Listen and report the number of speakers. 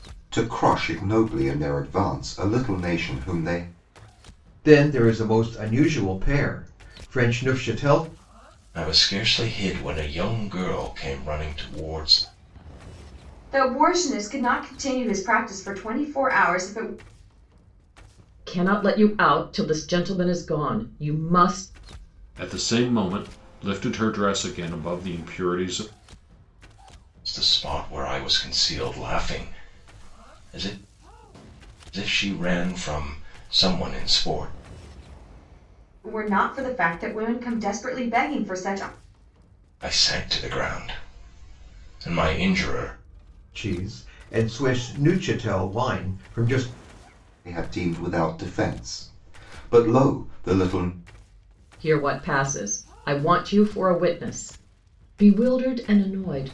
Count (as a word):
six